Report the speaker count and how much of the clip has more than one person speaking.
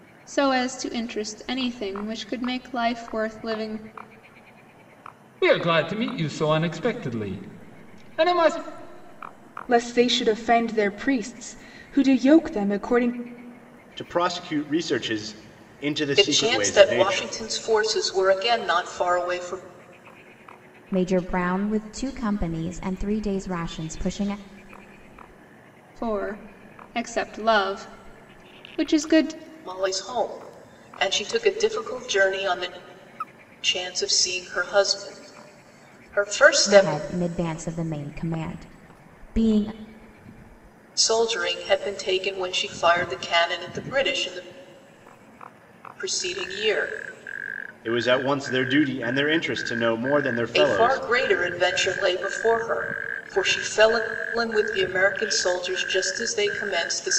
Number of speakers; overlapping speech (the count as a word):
six, about 4%